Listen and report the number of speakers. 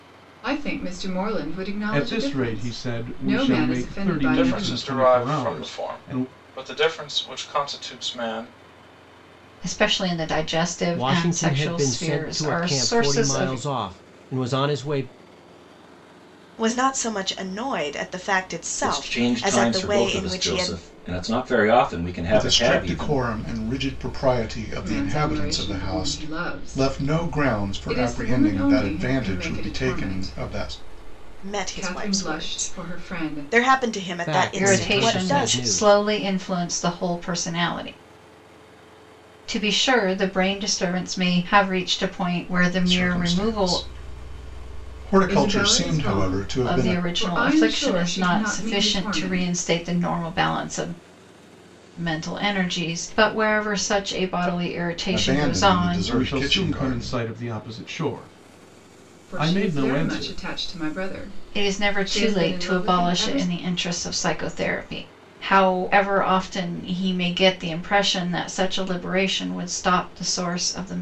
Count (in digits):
8